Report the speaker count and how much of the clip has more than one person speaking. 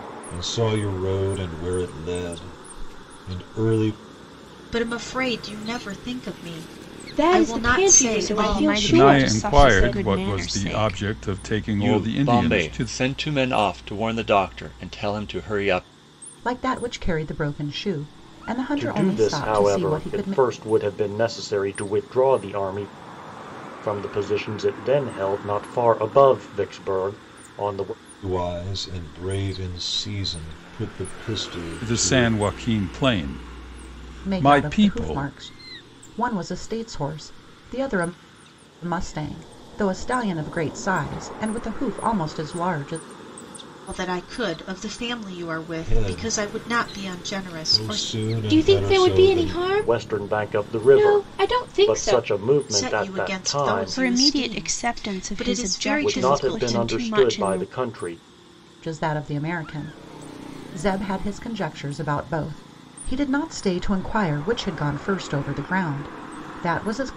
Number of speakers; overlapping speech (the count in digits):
8, about 29%